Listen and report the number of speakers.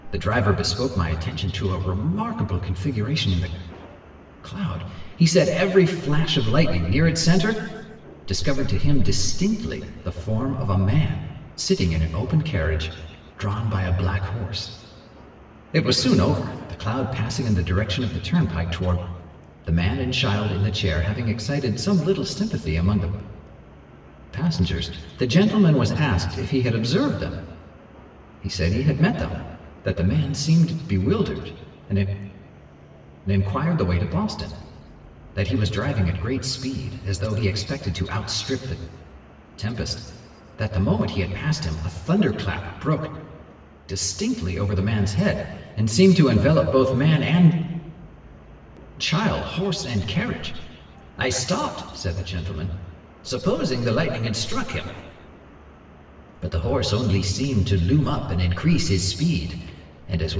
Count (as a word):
one